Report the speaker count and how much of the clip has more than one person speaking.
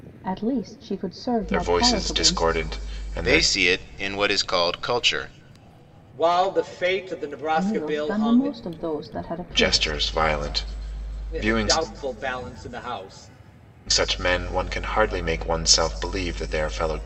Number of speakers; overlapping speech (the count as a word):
four, about 18%